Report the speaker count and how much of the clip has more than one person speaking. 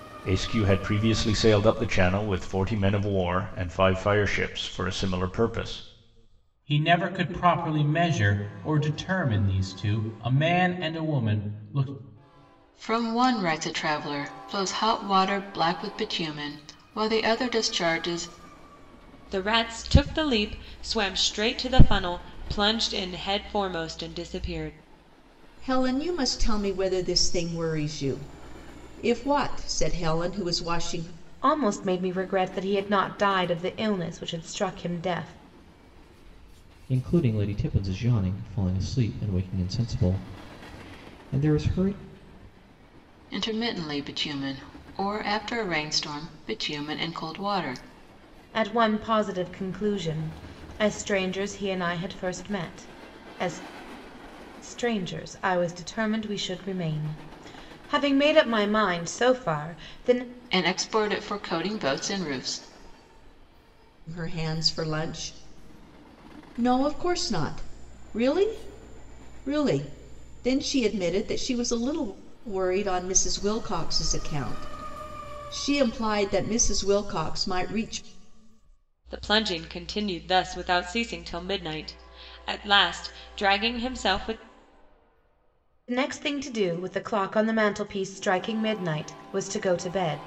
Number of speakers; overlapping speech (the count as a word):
seven, no overlap